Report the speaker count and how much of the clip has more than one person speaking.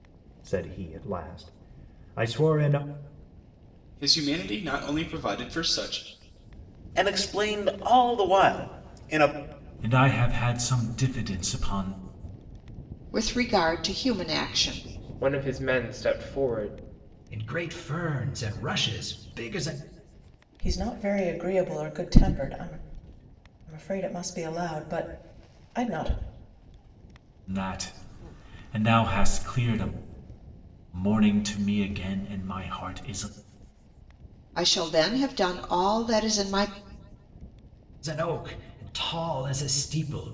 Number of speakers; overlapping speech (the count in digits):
8, no overlap